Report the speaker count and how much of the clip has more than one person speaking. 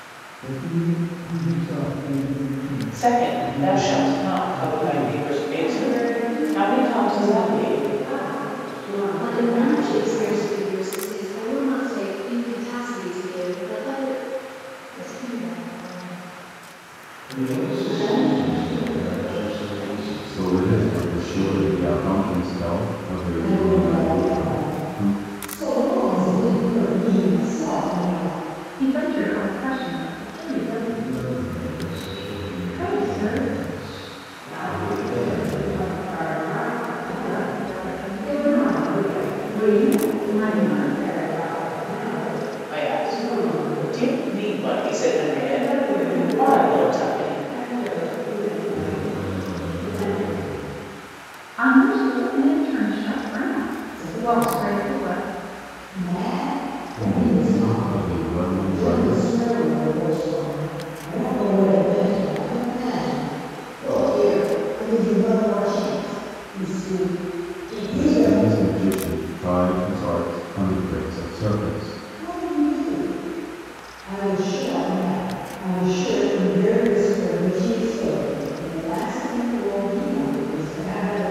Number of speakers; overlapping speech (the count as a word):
nine, about 37%